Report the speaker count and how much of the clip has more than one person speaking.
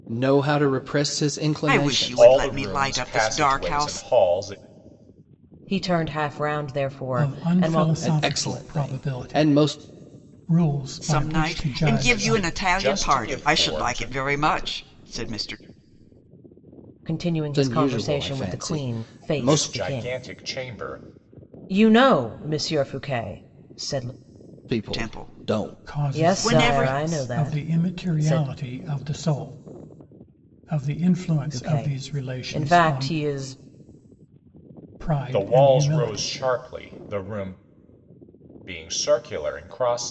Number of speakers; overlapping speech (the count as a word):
five, about 42%